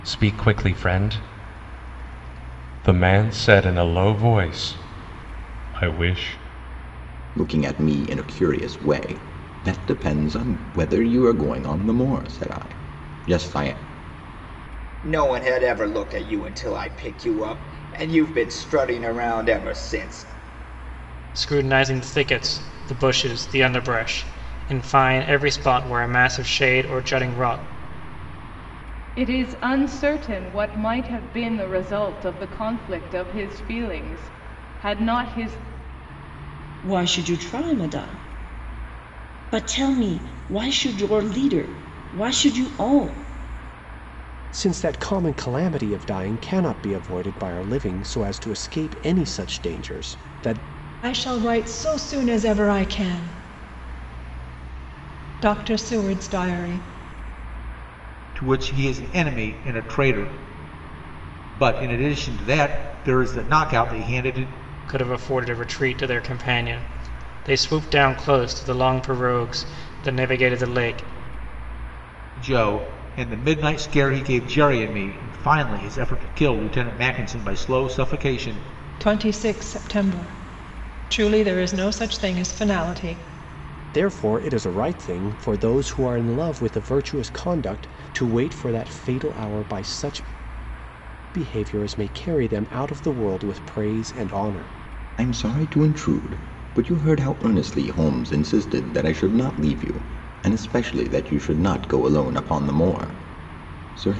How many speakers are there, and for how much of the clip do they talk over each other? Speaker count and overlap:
9, no overlap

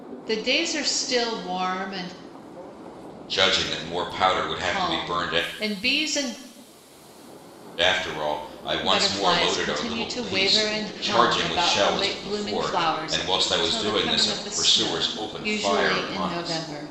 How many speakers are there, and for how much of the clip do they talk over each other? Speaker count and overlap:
2, about 48%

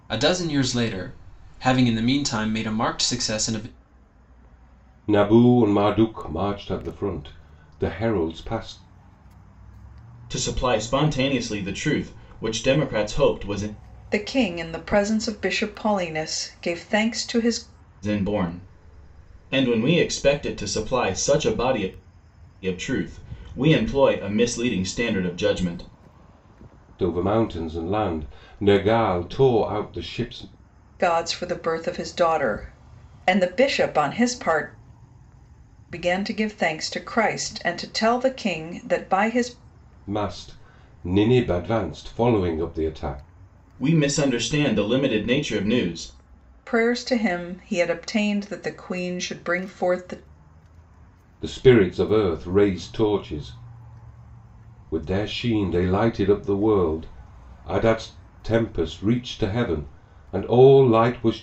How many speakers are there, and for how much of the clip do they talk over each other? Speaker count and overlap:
4, no overlap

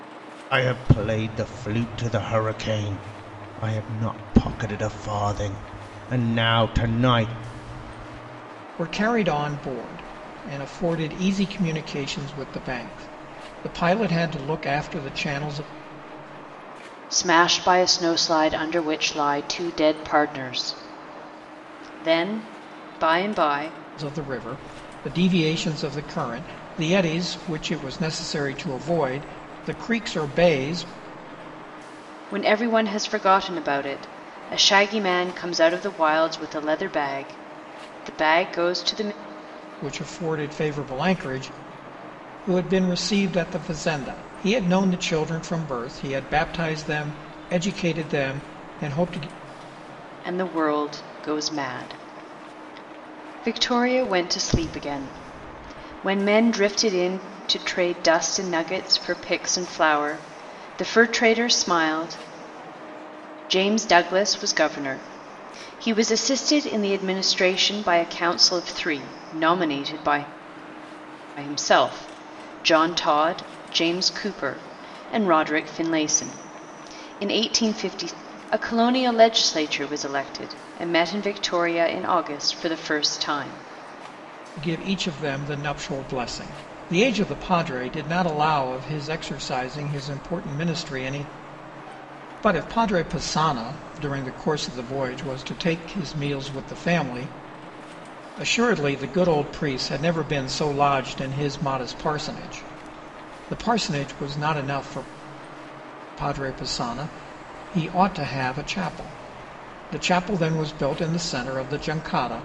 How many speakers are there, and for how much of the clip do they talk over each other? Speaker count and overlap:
3, no overlap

